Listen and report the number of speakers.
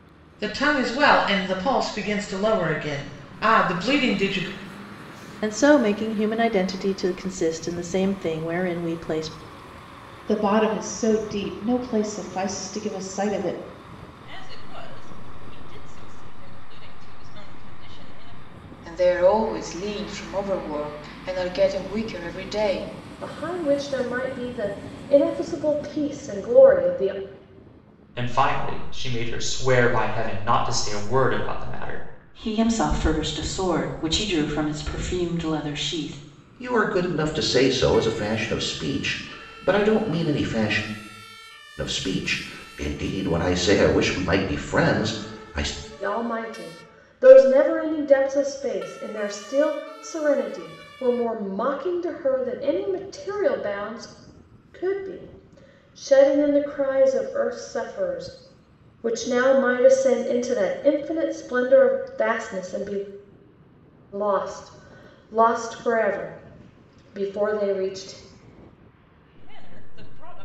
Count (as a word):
nine